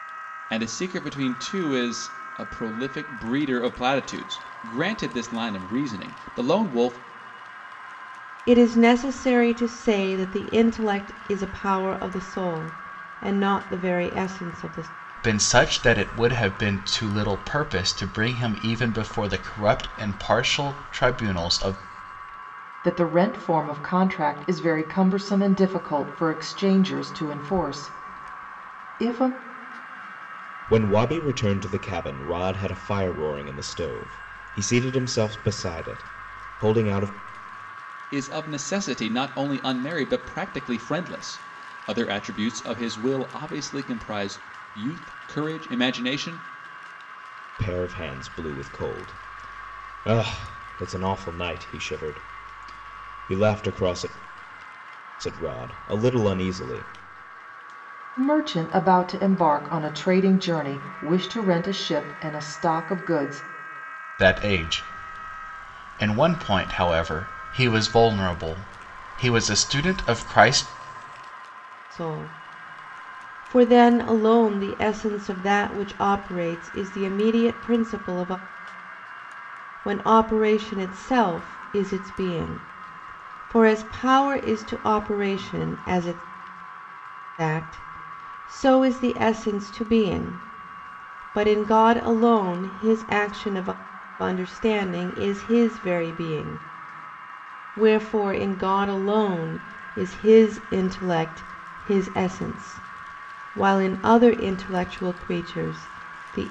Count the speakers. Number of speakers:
five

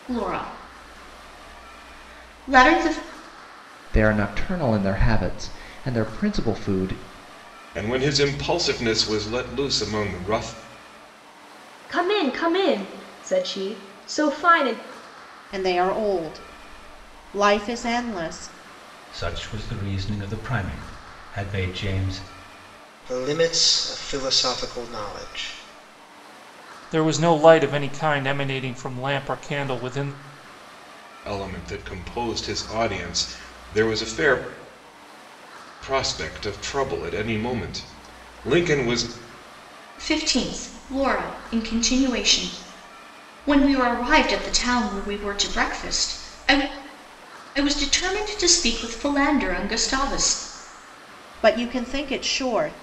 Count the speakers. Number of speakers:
eight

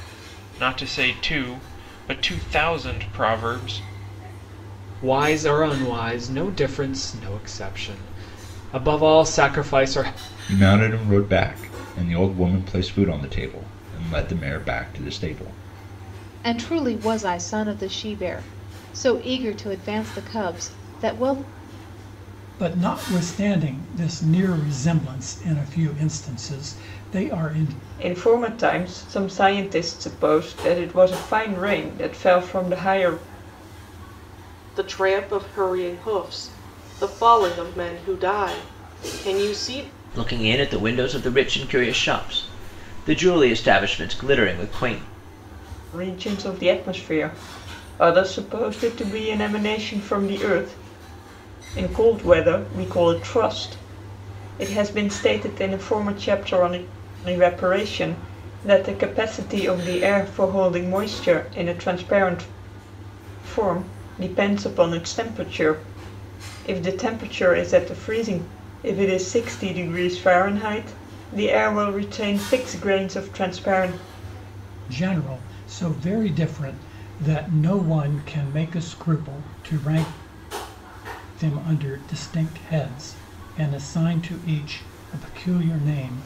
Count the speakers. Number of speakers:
eight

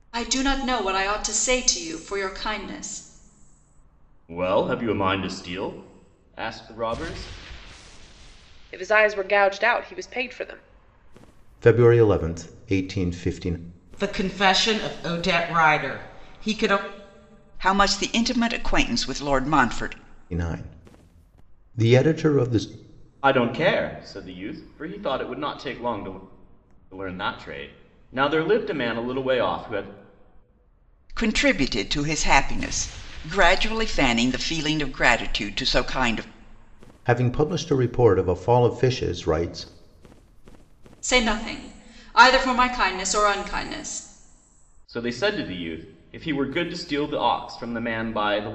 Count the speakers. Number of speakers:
six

